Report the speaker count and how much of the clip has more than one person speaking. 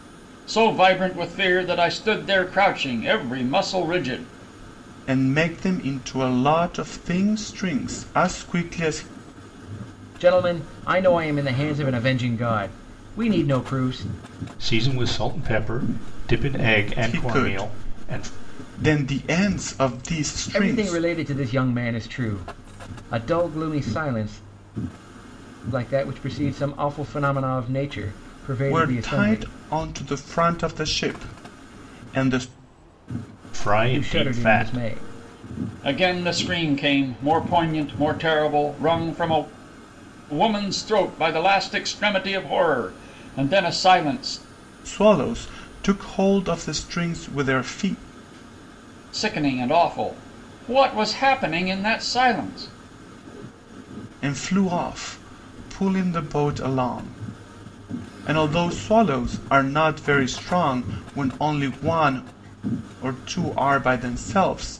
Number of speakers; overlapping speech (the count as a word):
four, about 6%